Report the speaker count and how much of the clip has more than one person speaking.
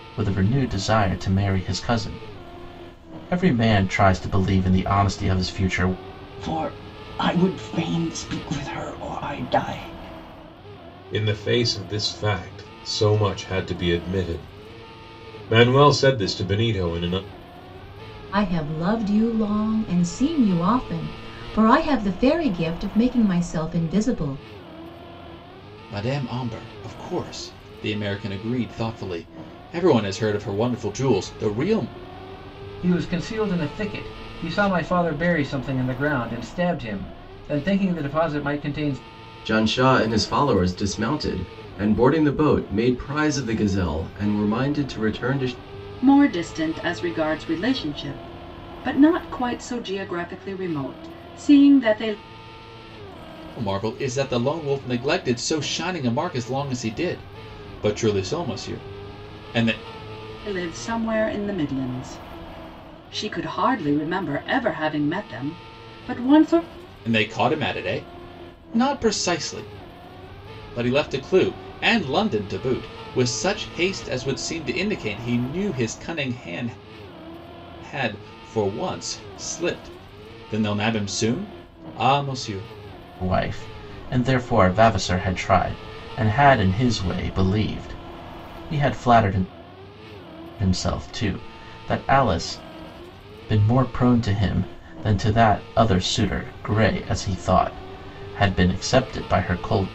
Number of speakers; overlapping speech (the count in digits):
8, no overlap